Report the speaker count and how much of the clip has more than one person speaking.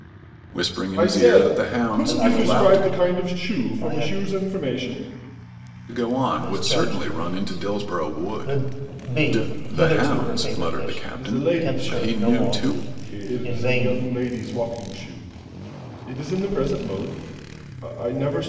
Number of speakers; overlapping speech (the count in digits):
3, about 57%